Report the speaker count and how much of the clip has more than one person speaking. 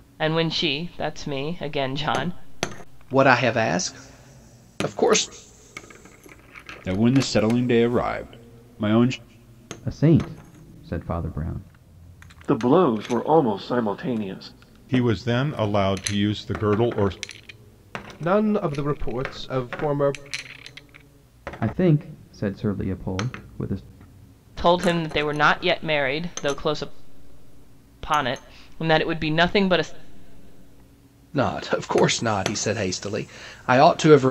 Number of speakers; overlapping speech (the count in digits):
7, no overlap